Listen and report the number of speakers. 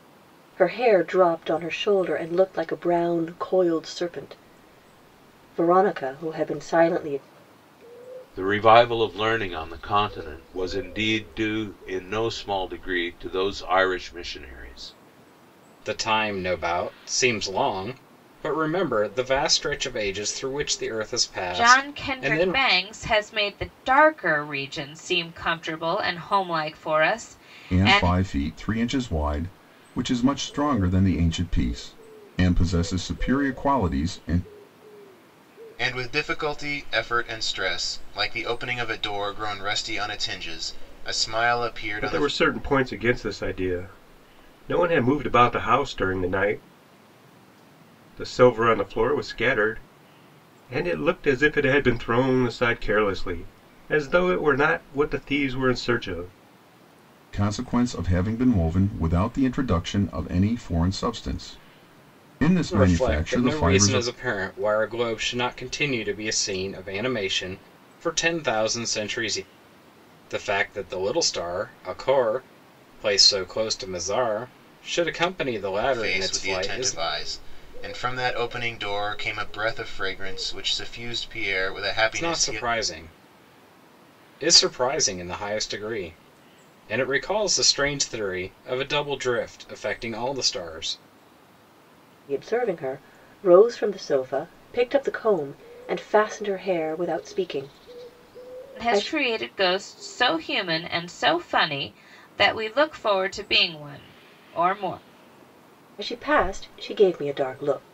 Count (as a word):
seven